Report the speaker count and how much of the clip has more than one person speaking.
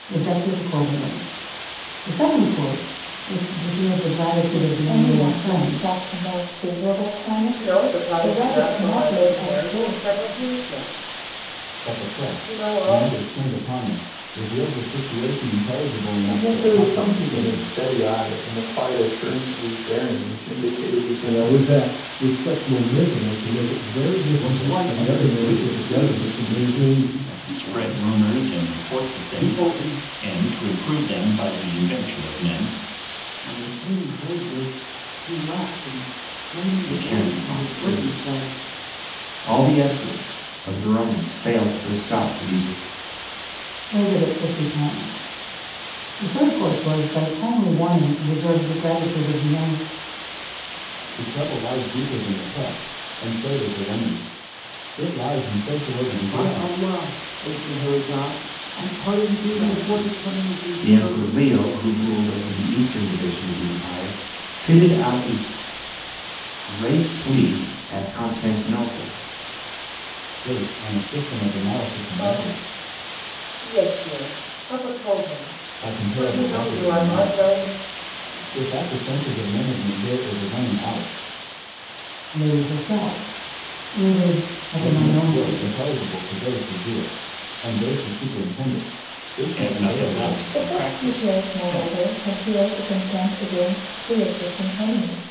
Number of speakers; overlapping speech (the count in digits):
10, about 25%